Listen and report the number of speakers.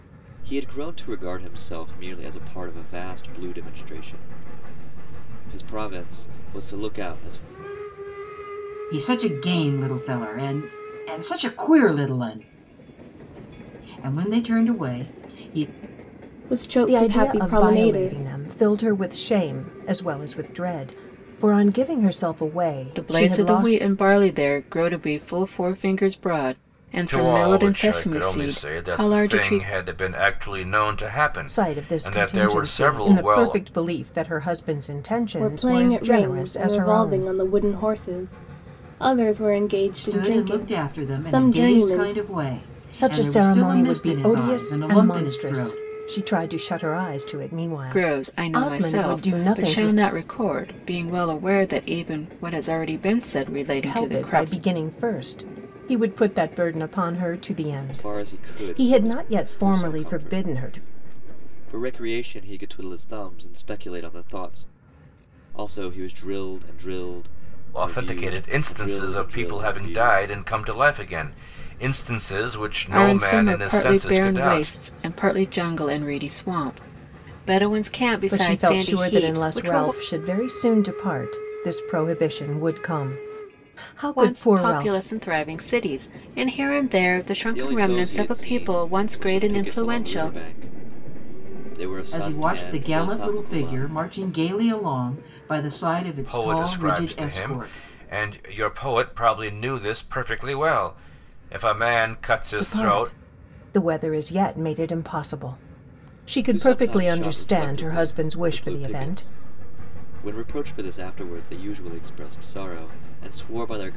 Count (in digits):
6